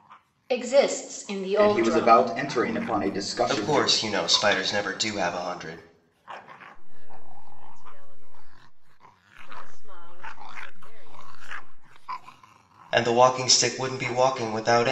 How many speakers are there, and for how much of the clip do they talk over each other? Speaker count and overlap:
four, about 8%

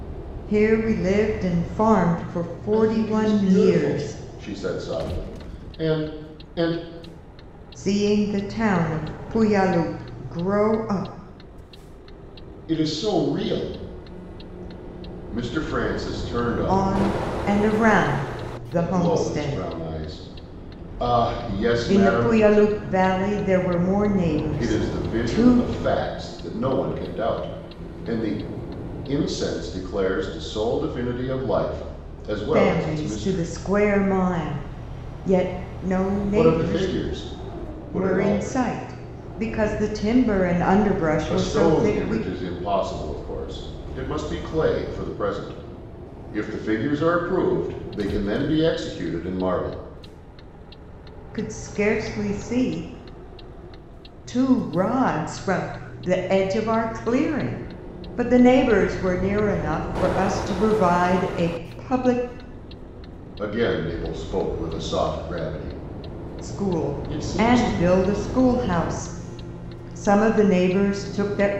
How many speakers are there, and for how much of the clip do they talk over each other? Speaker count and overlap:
two, about 13%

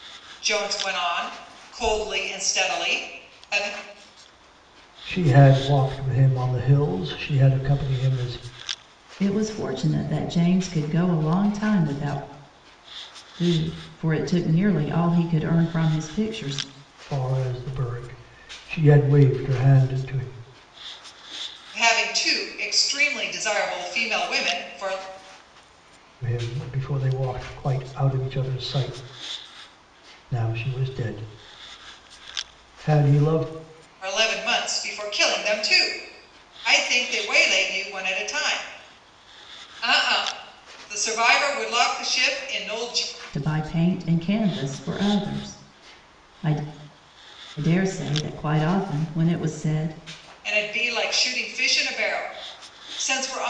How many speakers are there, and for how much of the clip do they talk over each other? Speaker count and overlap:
three, no overlap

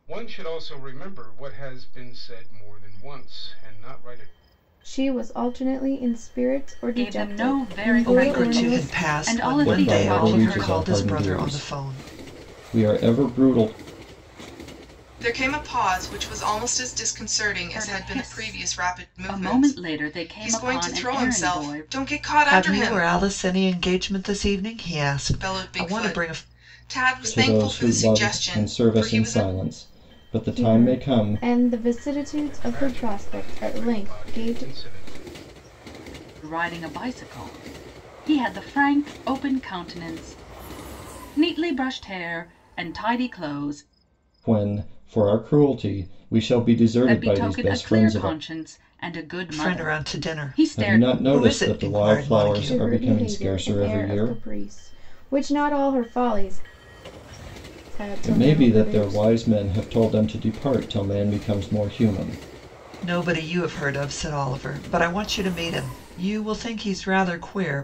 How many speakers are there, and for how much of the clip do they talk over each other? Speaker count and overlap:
six, about 35%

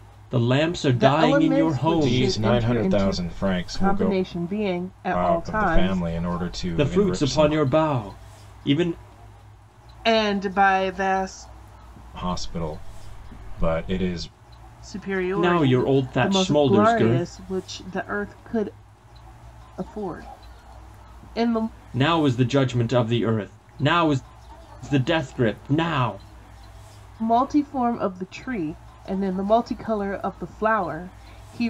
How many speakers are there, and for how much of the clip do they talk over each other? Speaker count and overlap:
three, about 21%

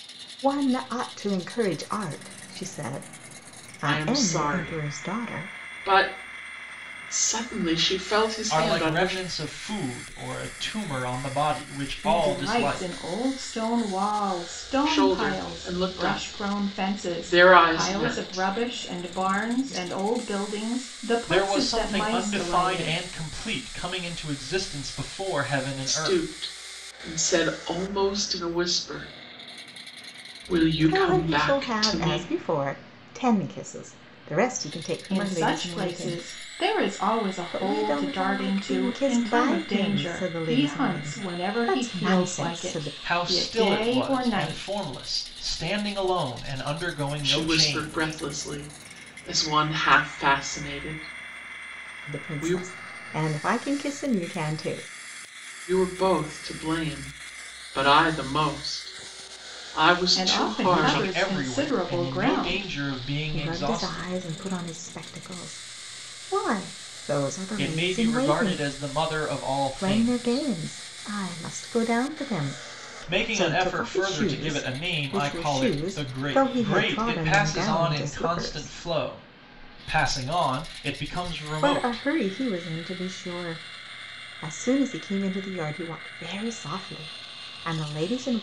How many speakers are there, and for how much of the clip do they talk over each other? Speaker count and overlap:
four, about 37%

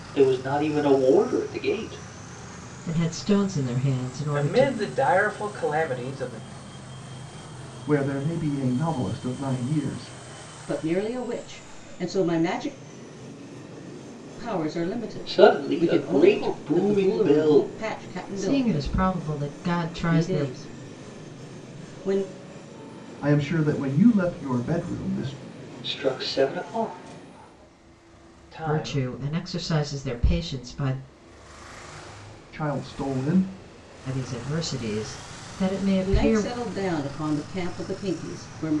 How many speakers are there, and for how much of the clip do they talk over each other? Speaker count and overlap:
five, about 12%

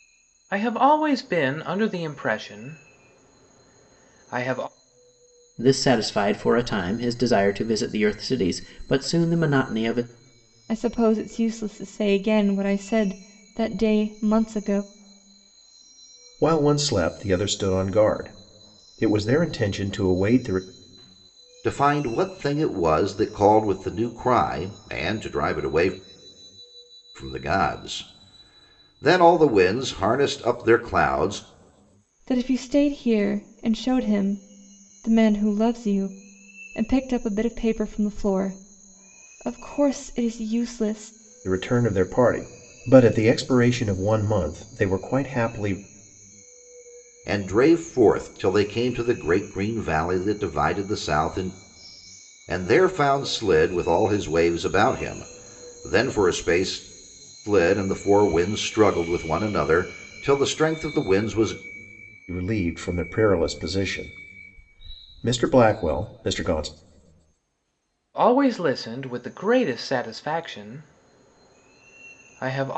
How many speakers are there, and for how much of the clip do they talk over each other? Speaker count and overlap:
five, no overlap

